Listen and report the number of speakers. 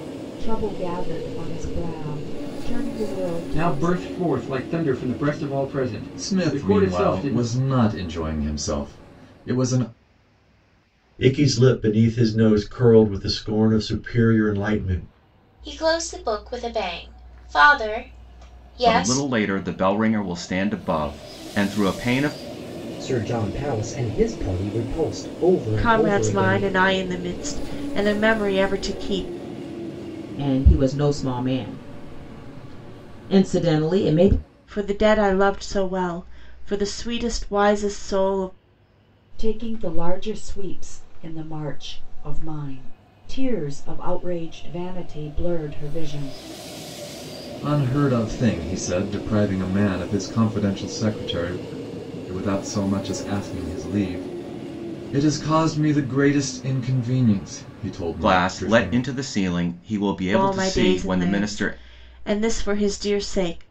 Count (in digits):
9